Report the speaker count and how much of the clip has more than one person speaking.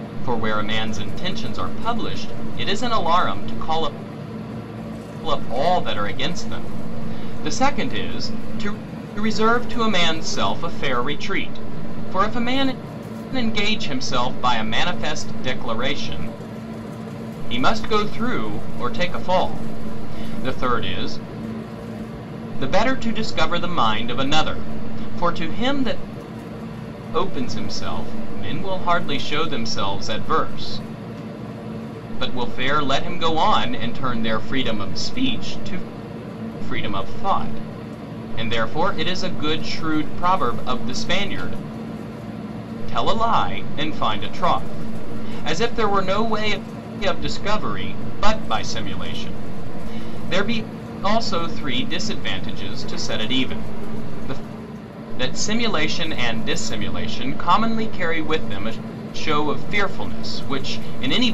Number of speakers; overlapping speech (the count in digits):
1, no overlap